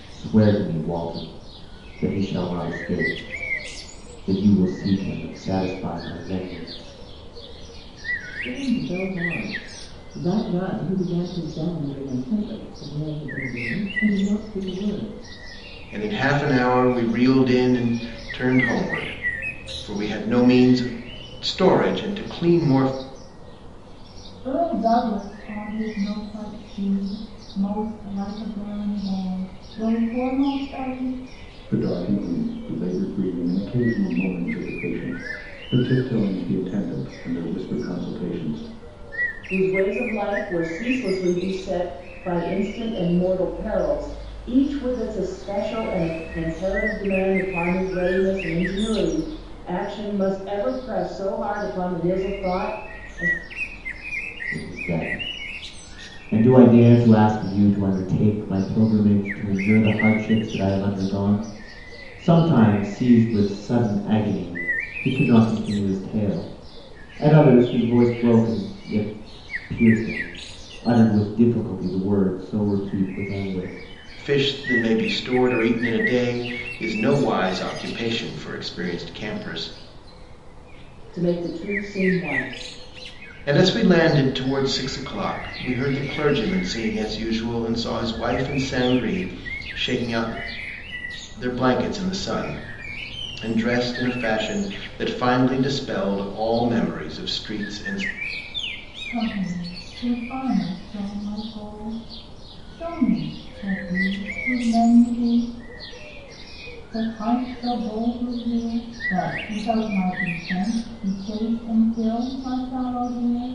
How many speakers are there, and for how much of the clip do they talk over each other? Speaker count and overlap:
six, no overlap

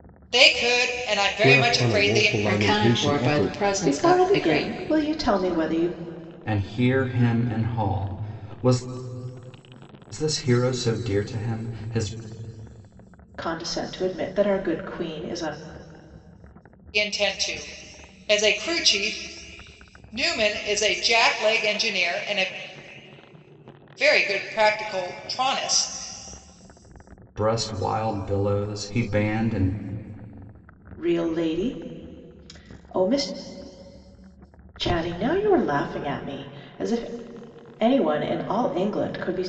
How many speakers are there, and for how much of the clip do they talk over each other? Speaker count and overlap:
five, about 8%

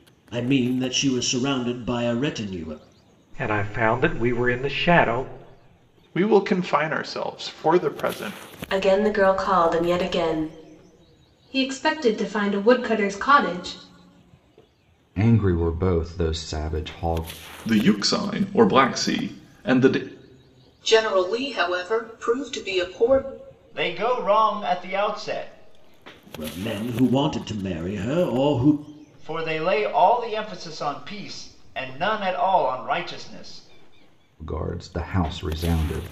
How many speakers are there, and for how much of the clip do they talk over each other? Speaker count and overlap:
nine, no overlap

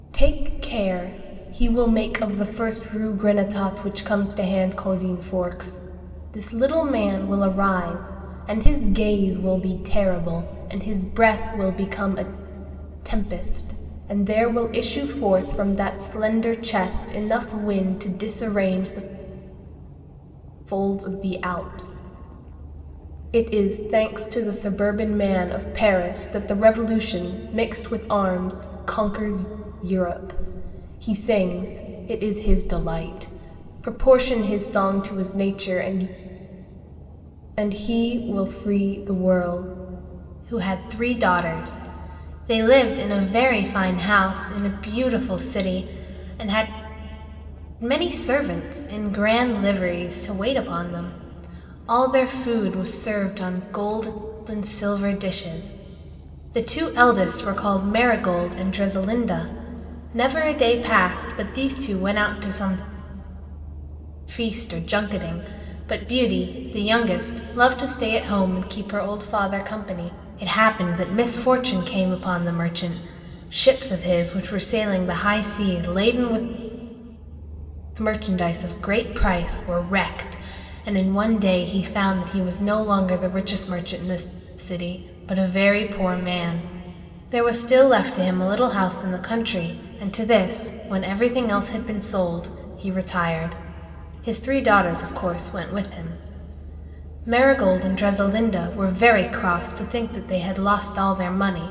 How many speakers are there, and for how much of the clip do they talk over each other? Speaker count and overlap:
one, no overlap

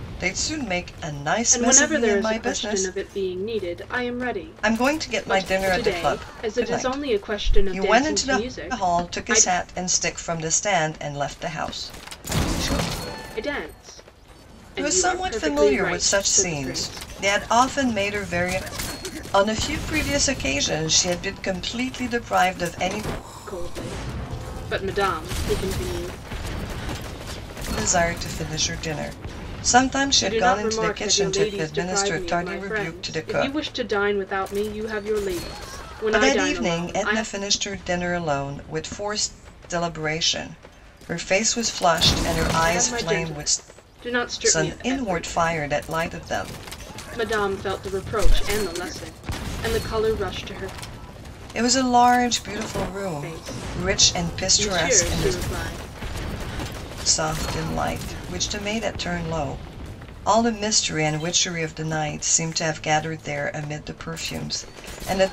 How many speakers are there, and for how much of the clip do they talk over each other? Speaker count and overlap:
two, about 26%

